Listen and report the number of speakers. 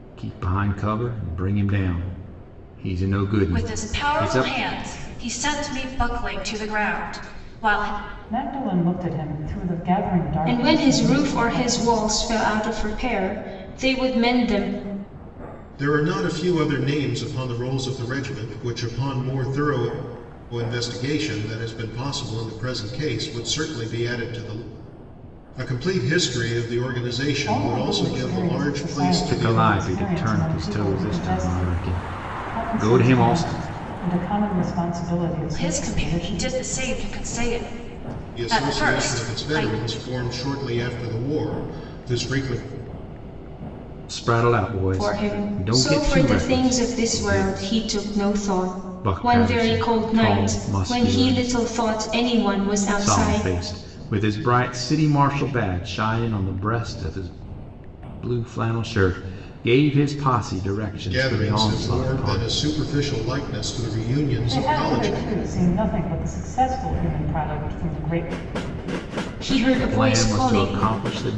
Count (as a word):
five